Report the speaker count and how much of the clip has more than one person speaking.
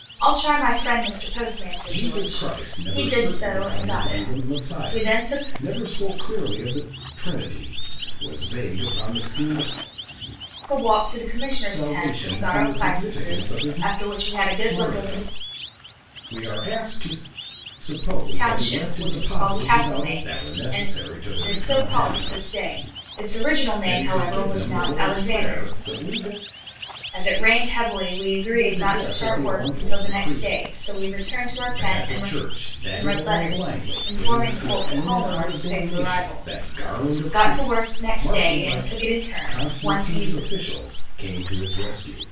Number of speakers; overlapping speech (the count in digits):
2, about 51%